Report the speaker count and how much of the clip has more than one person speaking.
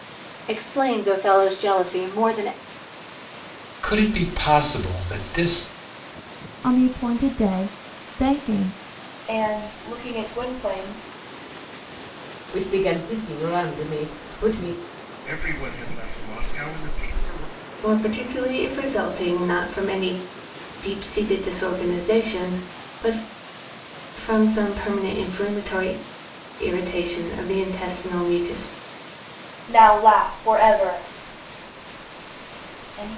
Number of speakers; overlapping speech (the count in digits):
7, no overlap